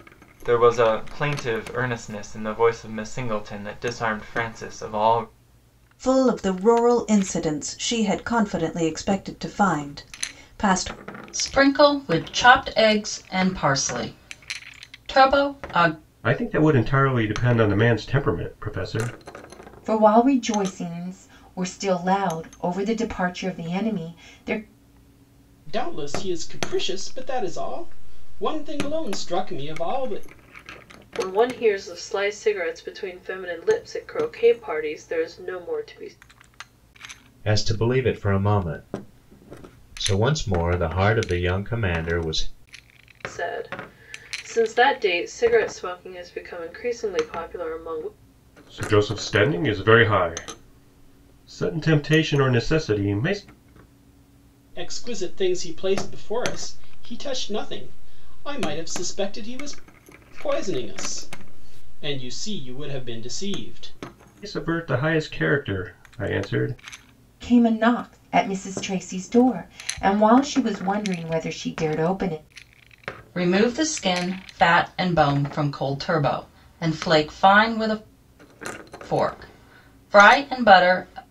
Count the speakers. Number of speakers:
8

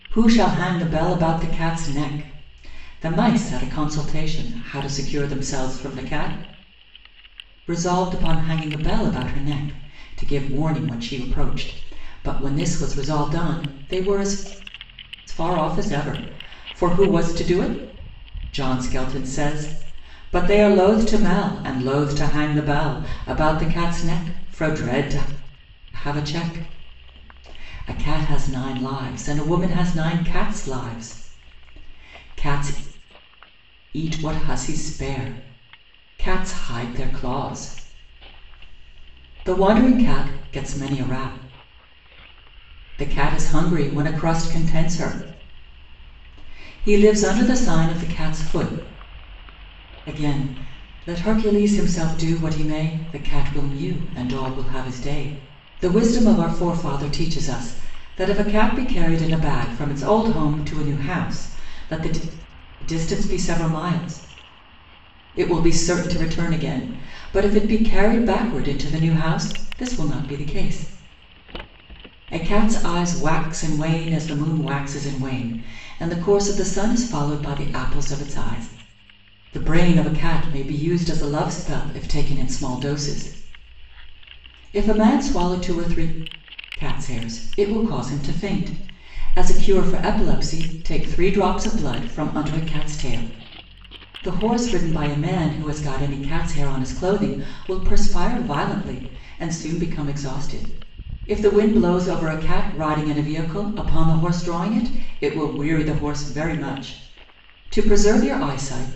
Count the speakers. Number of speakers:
1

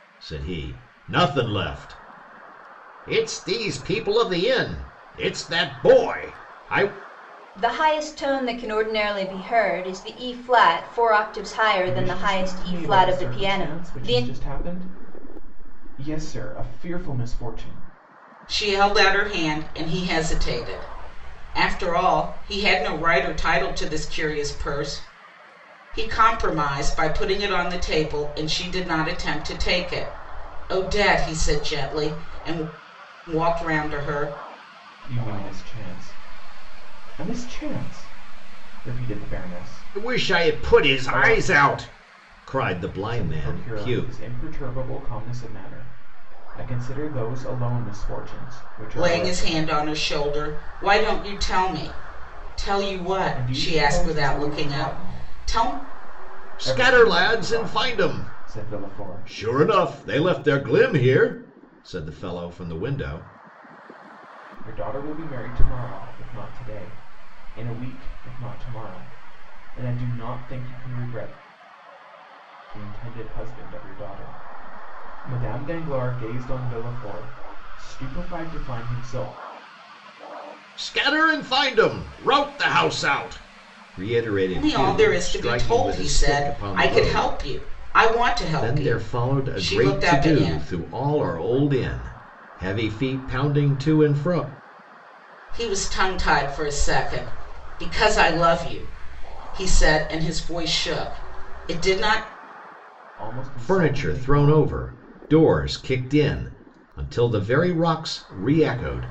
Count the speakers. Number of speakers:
4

